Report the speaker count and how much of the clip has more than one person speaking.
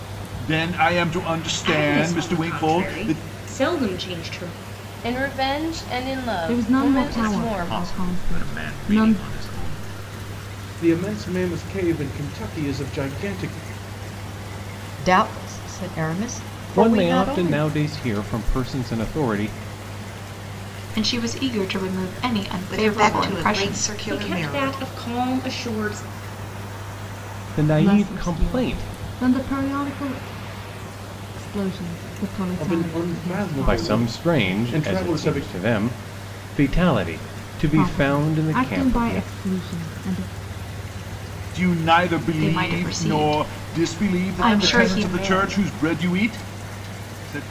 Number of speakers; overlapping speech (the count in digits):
10, about 34%